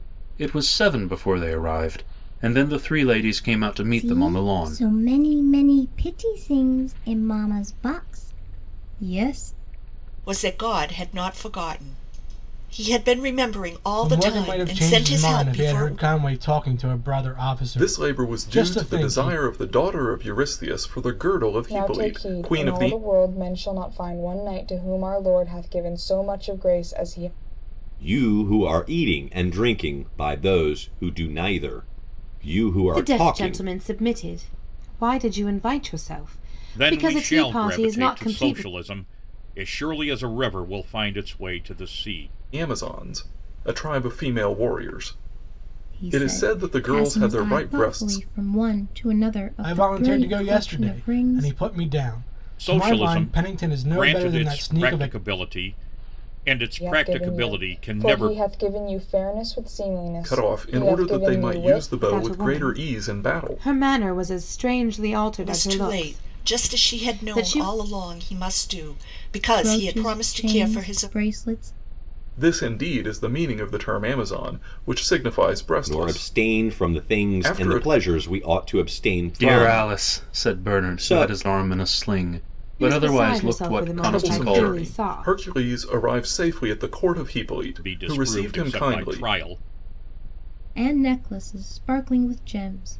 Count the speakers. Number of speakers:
nine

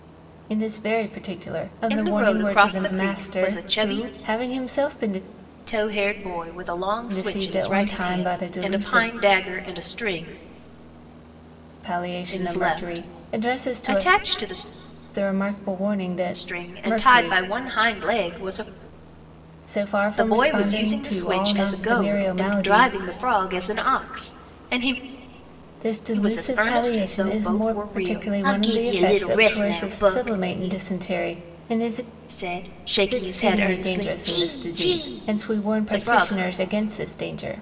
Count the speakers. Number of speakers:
two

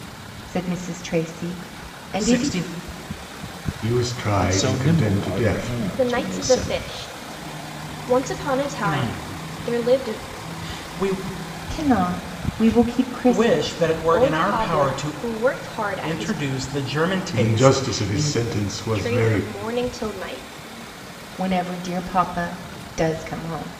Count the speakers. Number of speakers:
five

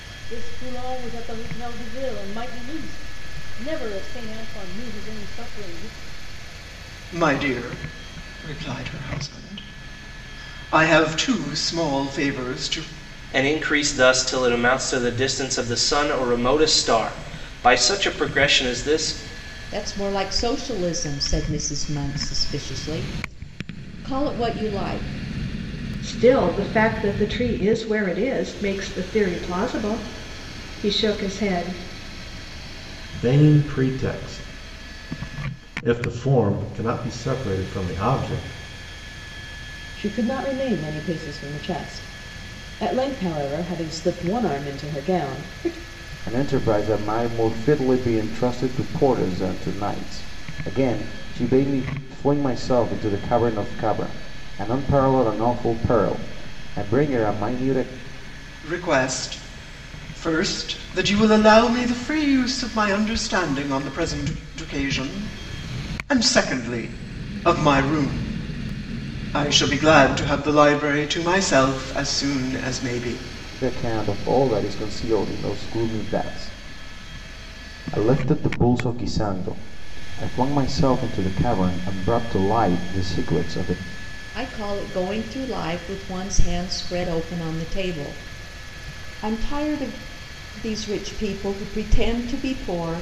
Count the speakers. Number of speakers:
eight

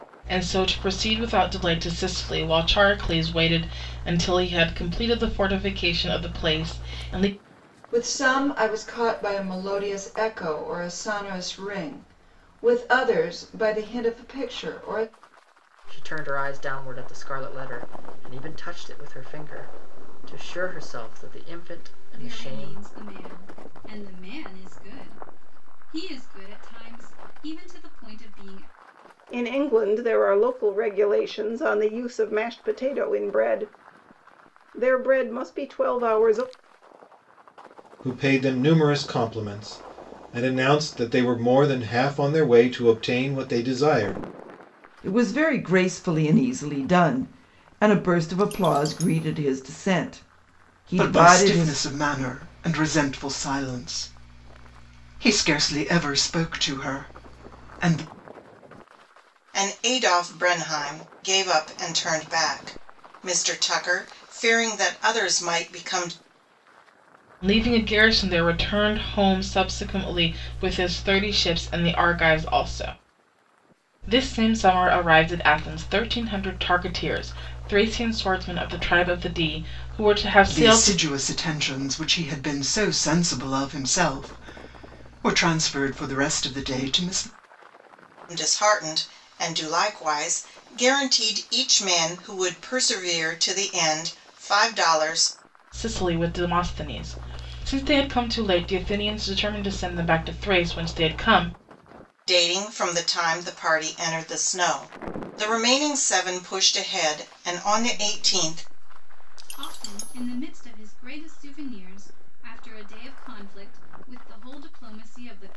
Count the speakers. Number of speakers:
nine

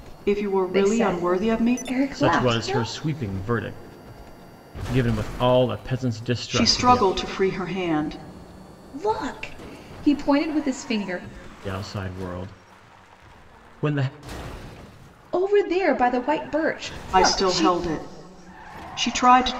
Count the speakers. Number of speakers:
three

